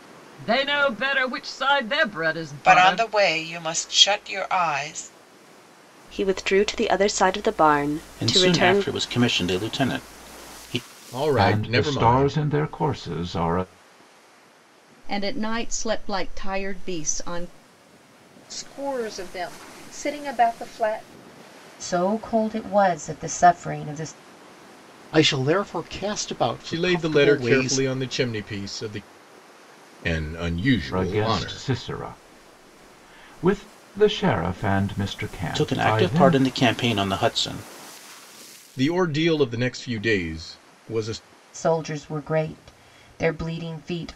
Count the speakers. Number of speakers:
10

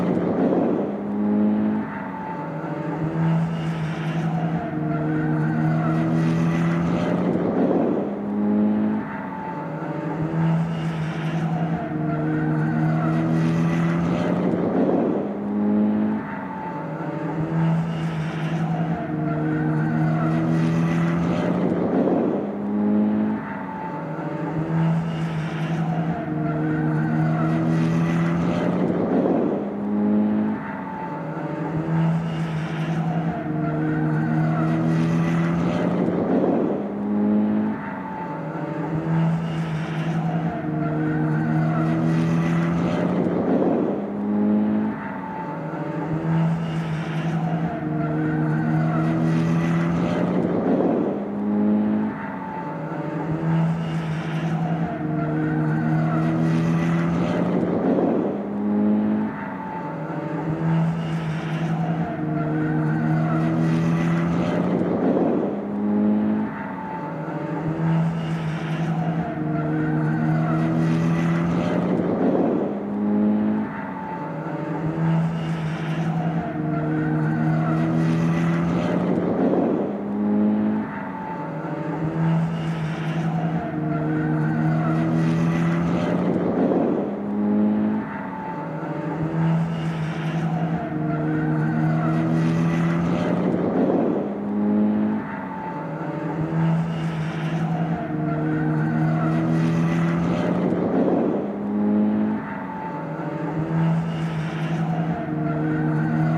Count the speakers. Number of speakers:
0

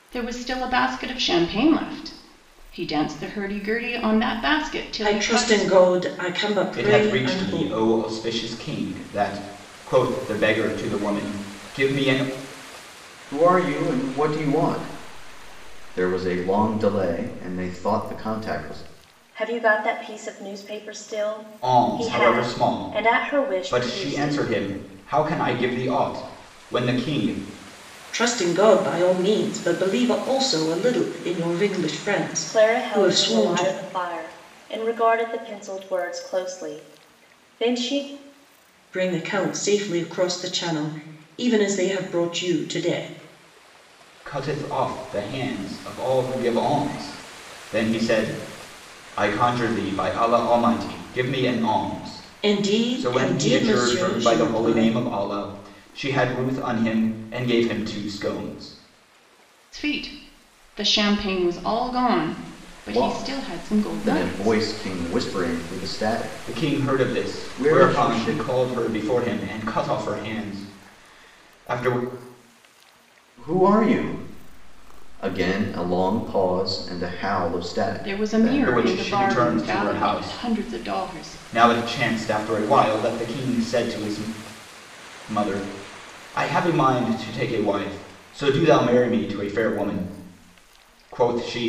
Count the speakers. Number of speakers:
5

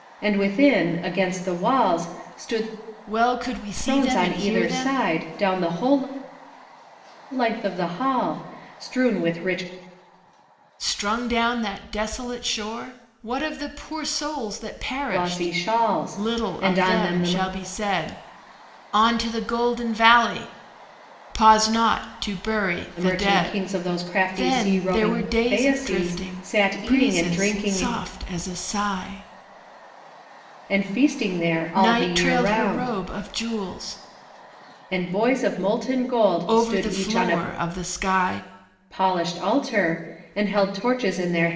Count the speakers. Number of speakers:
2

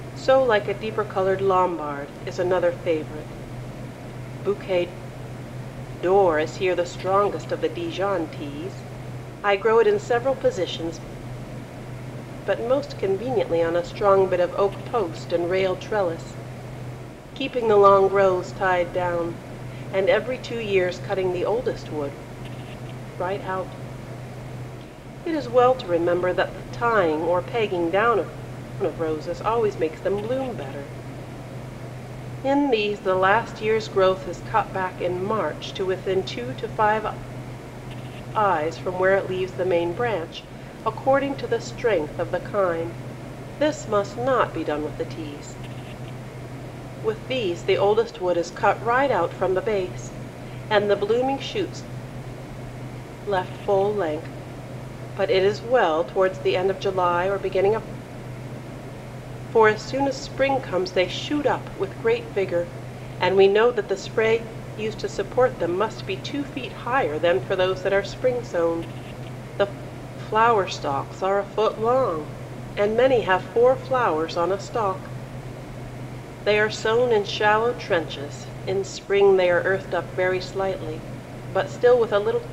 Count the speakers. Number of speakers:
1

